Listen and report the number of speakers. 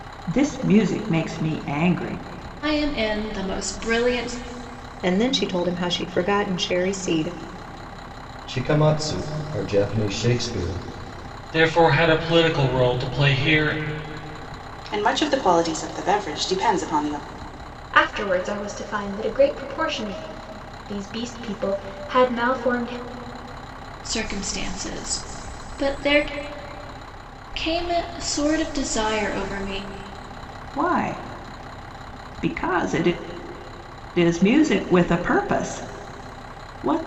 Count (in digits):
7